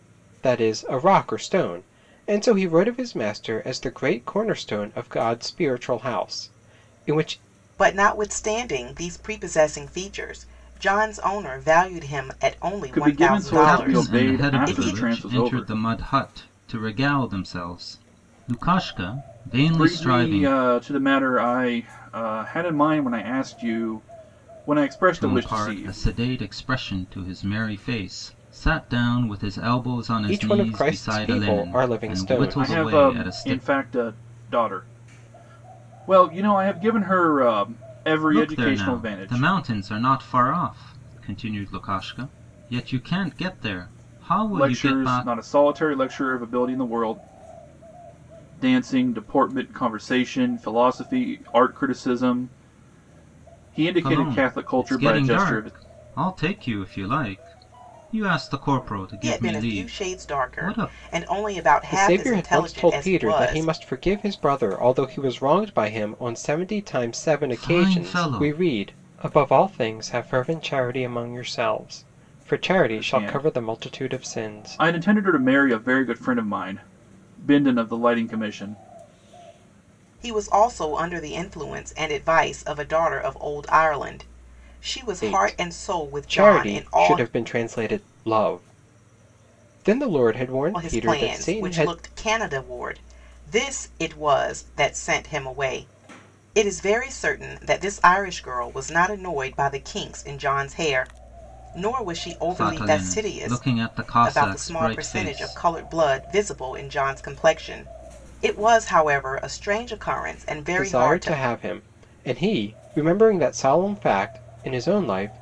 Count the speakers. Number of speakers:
four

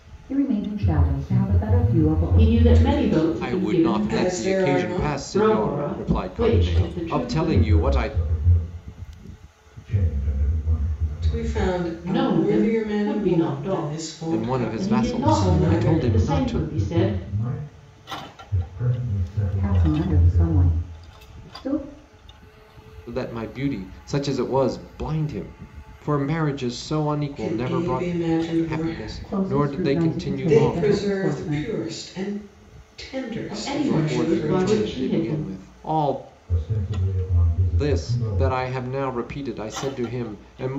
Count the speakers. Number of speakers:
five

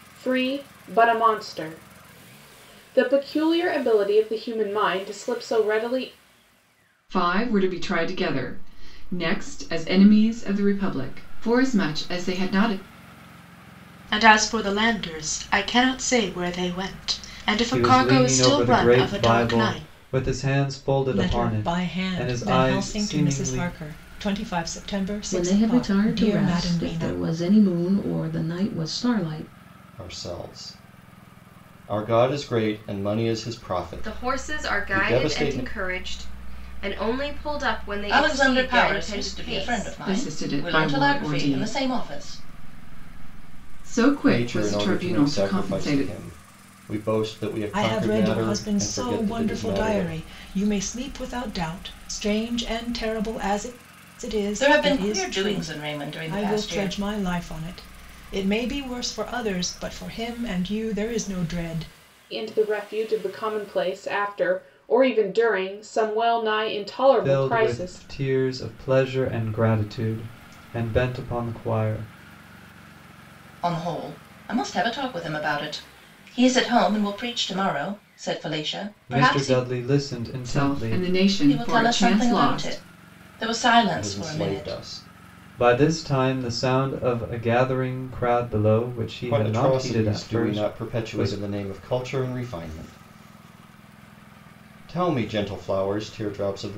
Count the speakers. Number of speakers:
nine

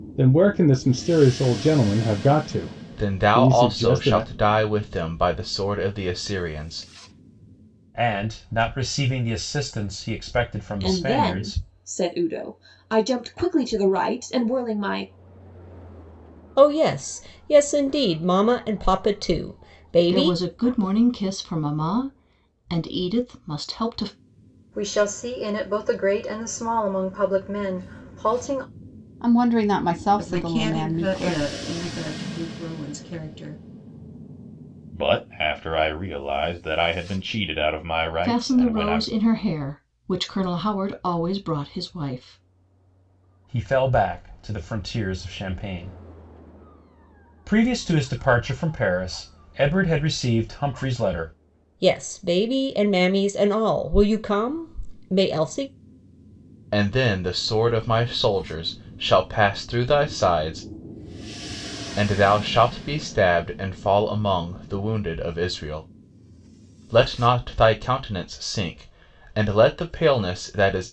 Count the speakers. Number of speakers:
ten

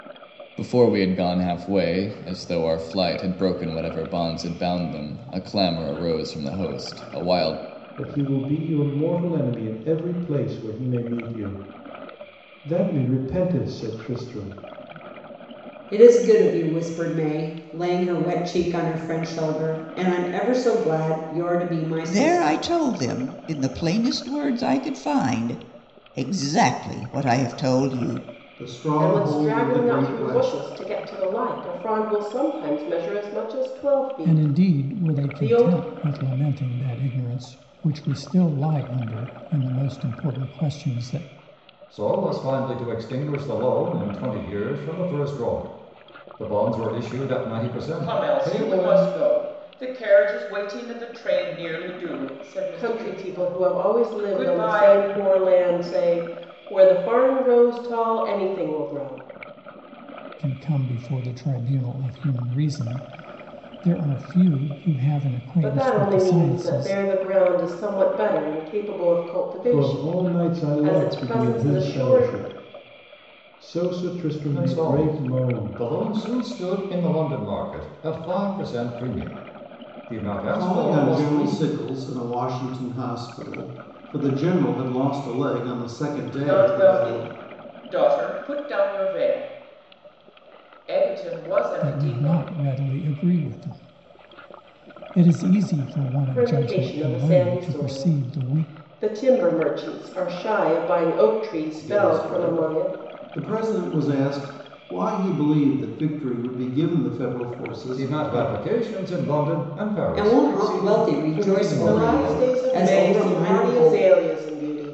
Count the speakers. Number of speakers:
nine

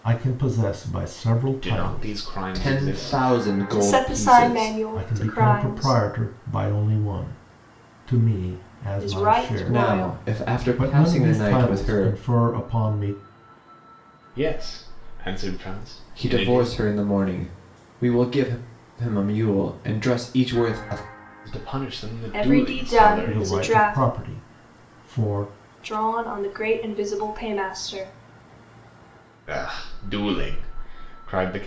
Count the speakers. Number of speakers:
four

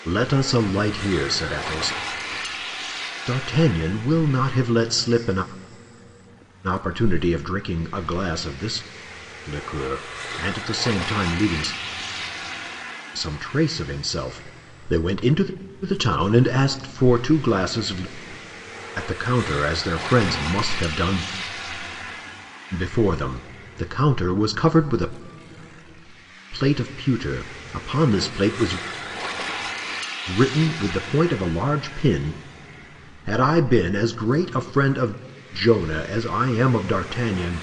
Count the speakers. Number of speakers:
one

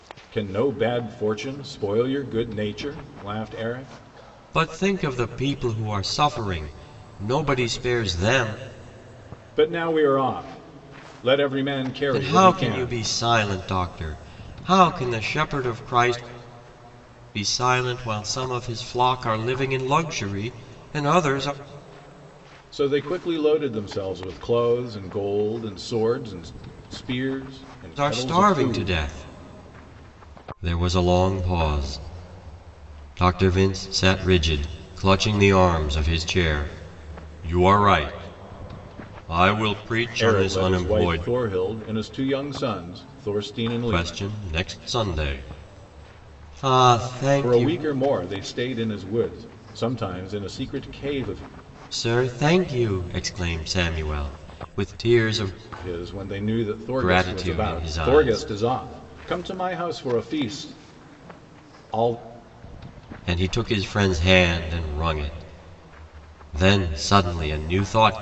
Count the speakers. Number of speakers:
two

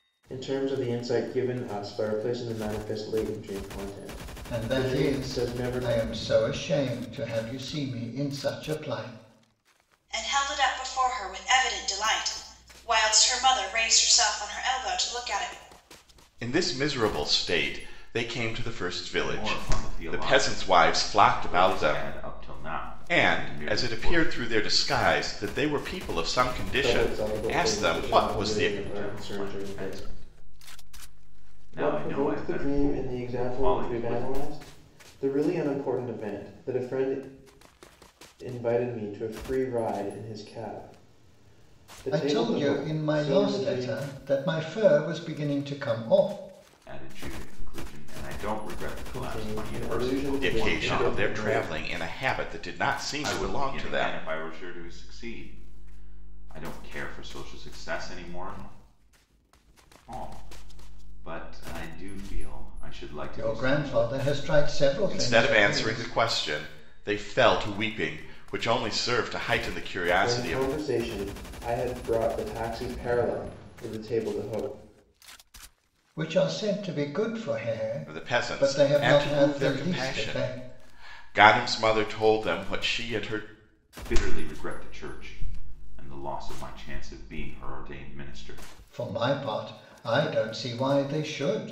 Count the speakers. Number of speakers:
five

